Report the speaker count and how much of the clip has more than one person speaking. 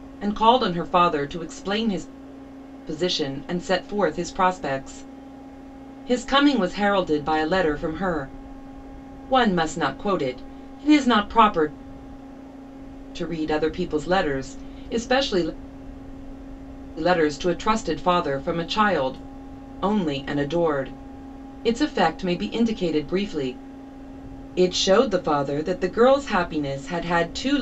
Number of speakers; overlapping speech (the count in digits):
1, no overlap